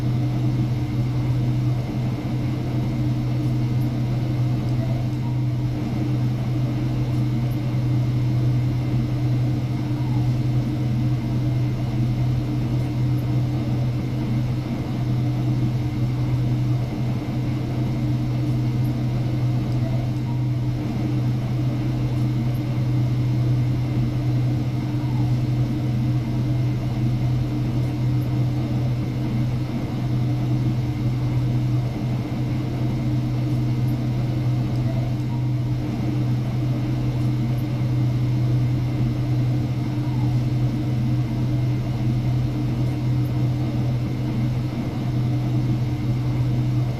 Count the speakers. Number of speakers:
0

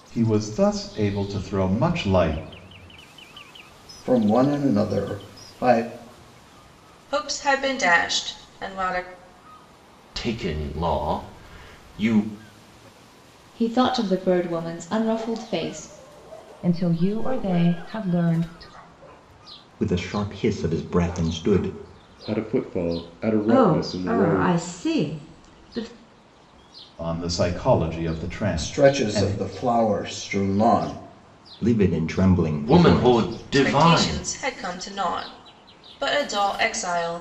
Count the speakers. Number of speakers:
9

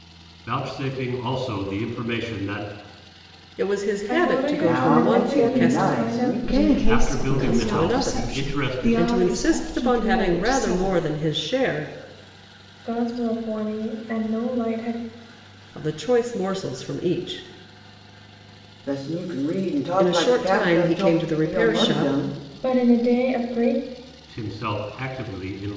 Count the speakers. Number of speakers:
5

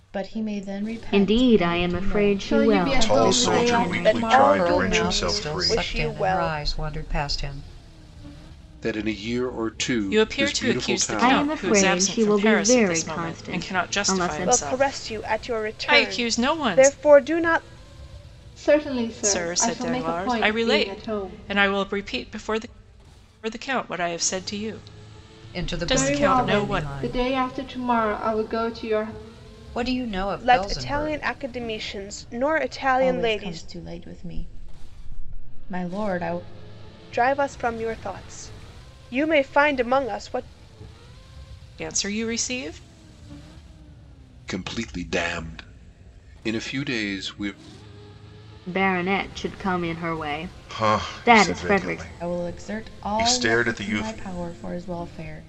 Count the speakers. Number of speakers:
8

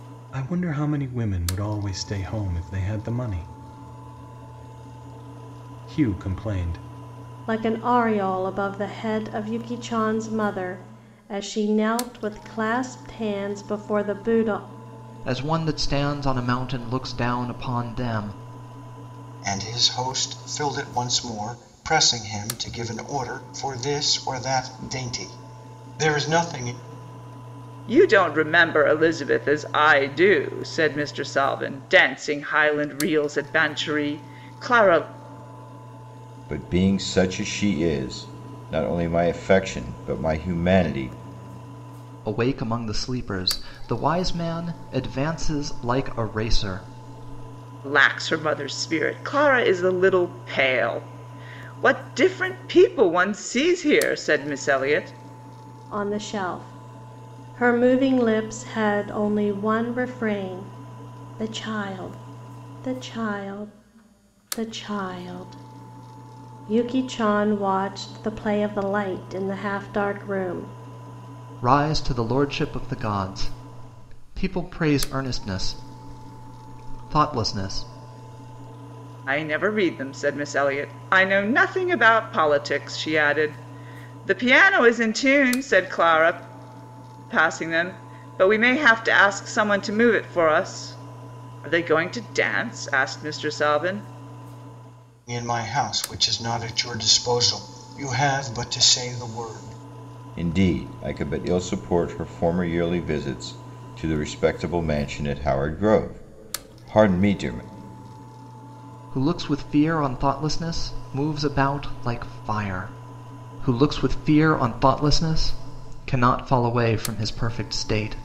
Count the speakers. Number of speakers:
6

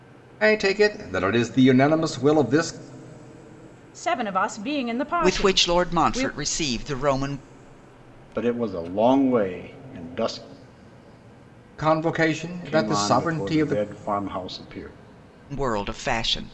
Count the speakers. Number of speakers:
4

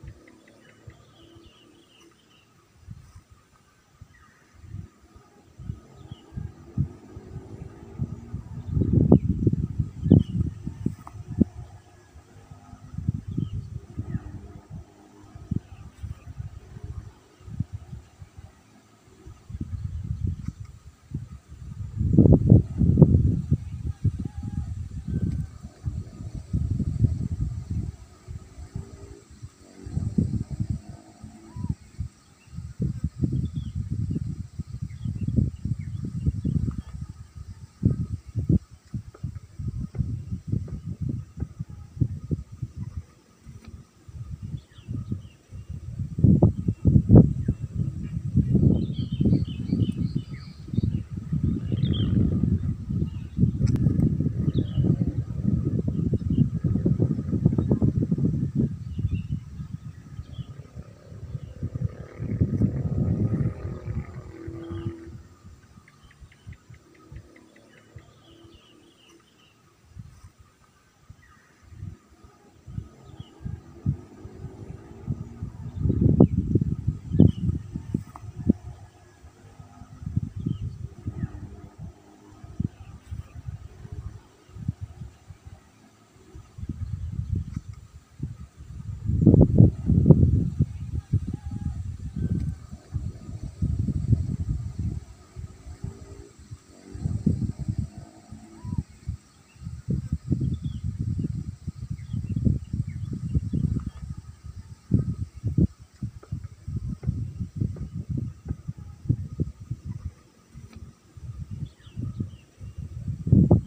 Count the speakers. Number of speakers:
0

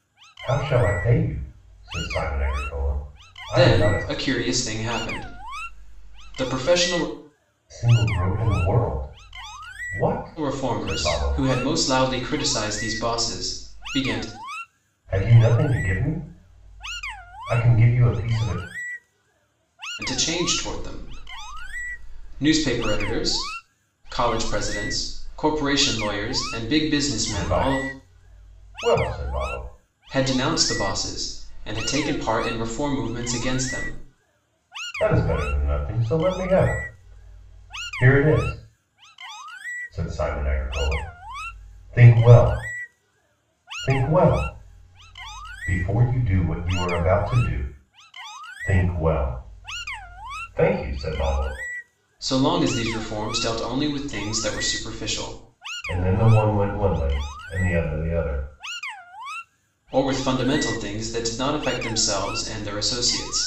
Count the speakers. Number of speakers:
2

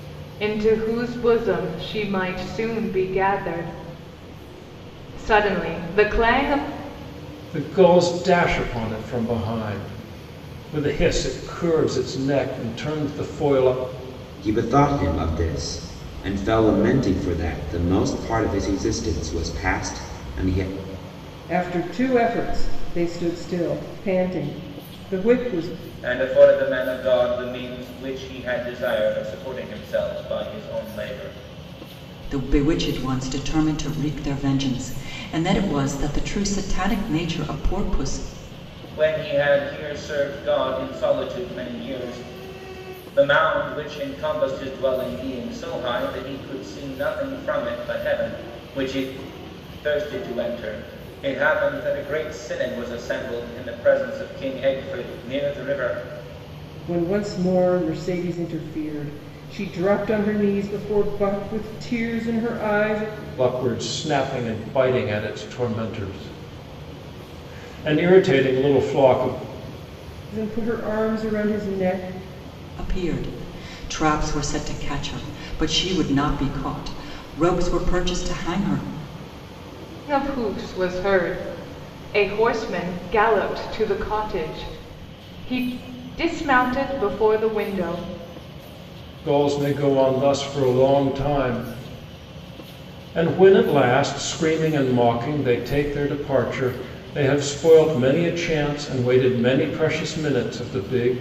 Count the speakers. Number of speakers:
6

